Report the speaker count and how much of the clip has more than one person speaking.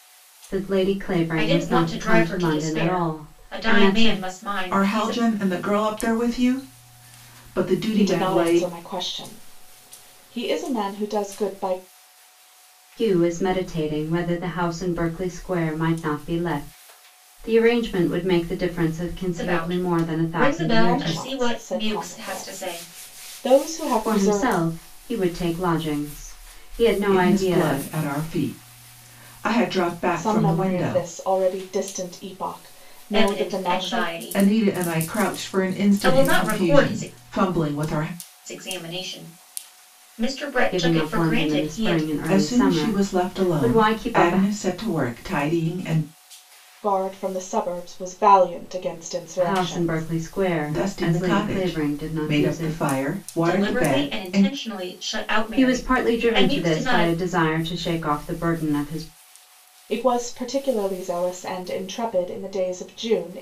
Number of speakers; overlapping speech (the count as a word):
four, about 37%